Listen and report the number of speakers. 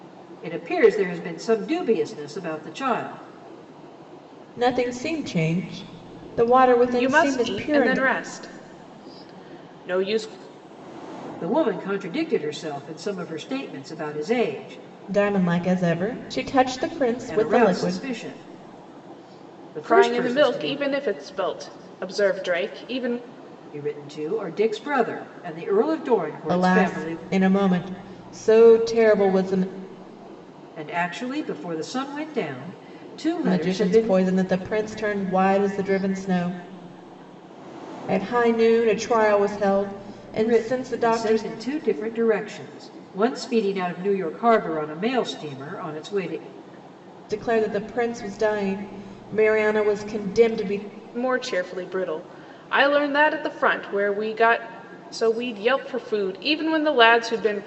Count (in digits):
3